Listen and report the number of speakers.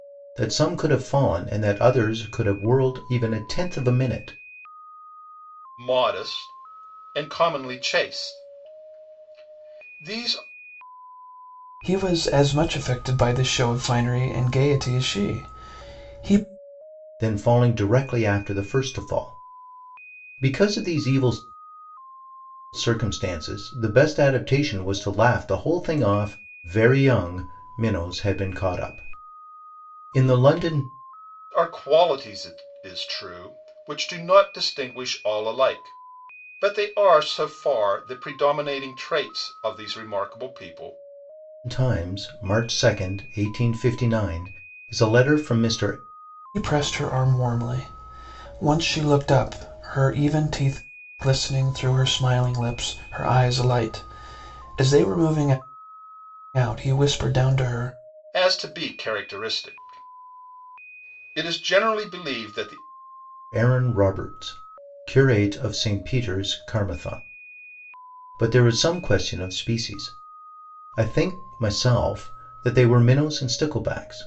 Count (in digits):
3